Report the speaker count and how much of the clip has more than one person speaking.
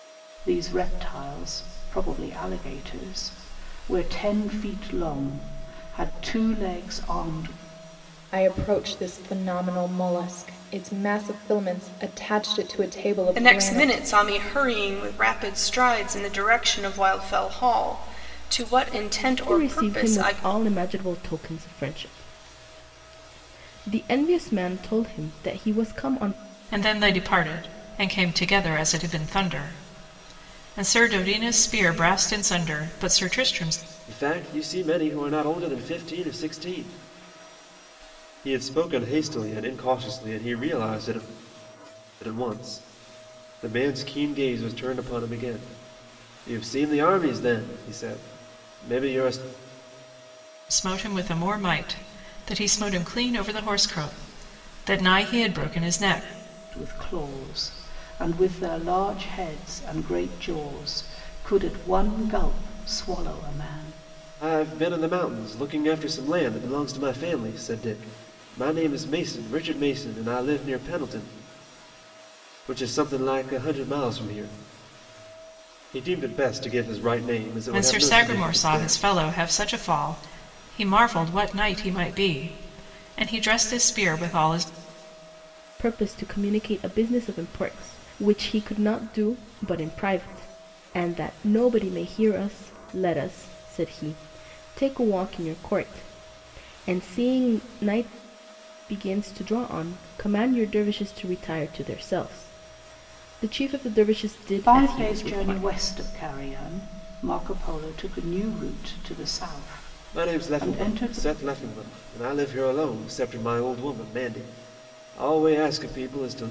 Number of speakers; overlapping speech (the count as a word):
six, about 5%